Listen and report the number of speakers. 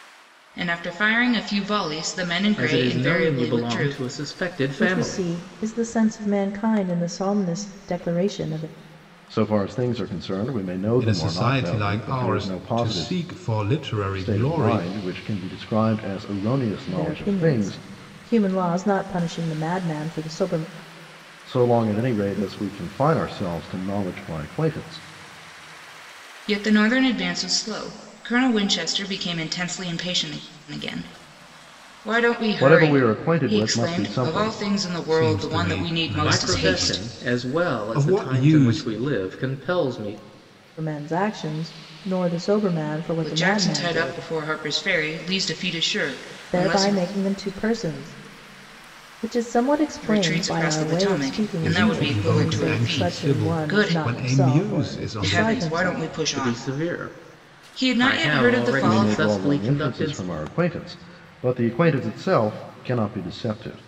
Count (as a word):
five